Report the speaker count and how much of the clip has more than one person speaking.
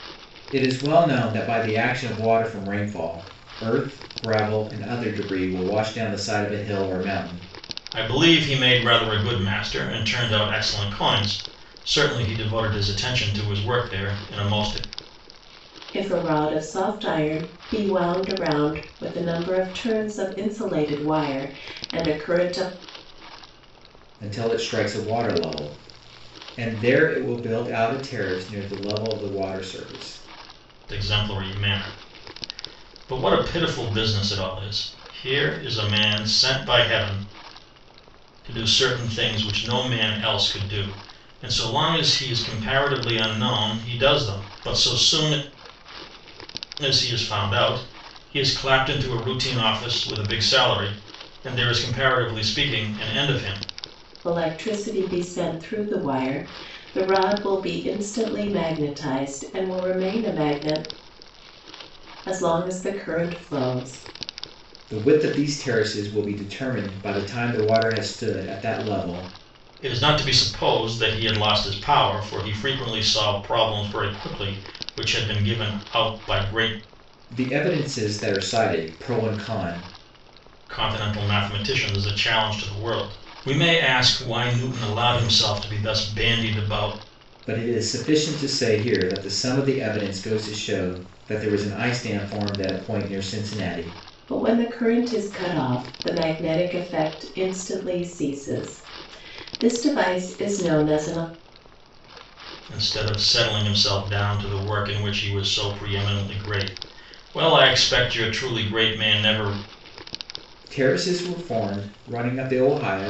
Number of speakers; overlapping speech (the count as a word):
three, no overlap